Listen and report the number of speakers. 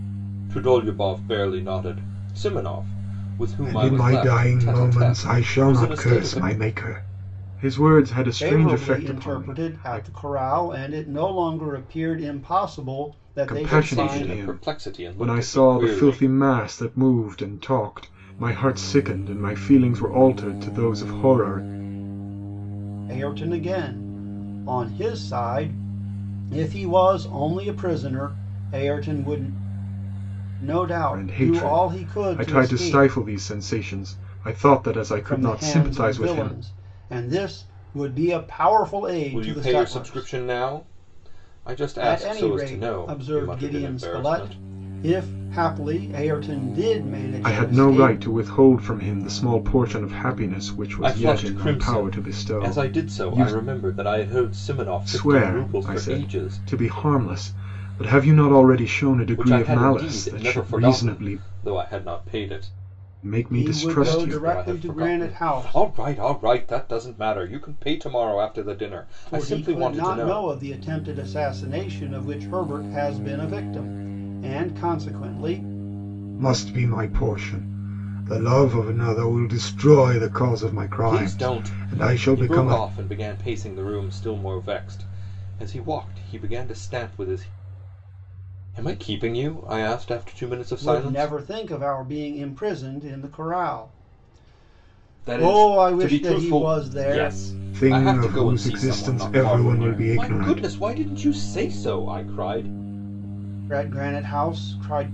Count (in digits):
3